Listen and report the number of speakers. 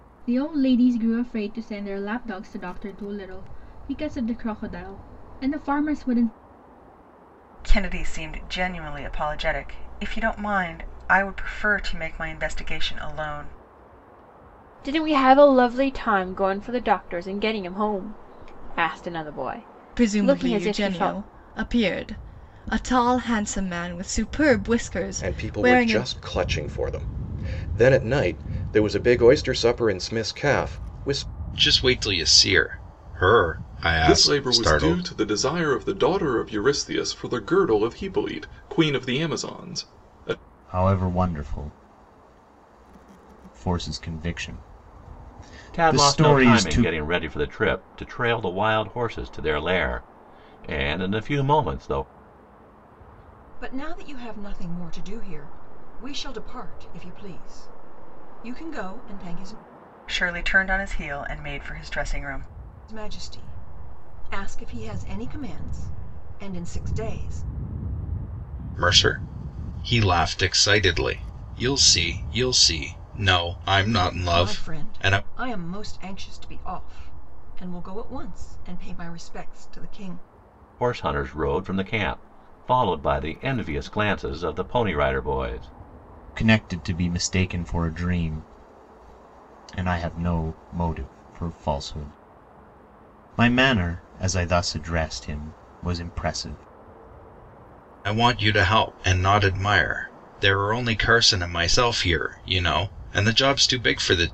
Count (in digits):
10